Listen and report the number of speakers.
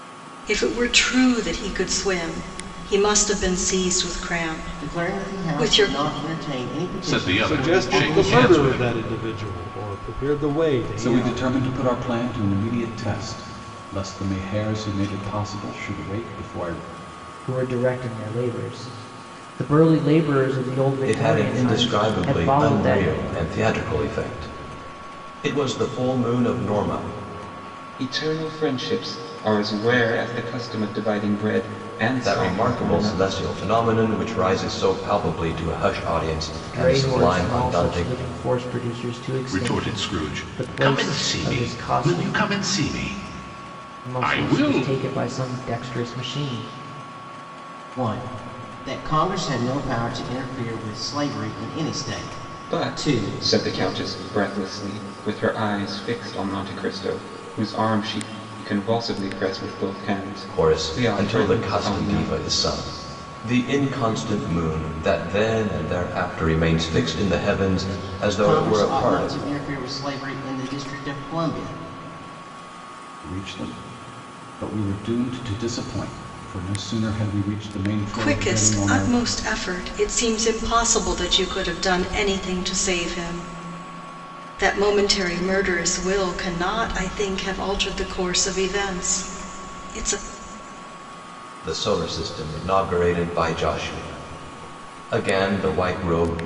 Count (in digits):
8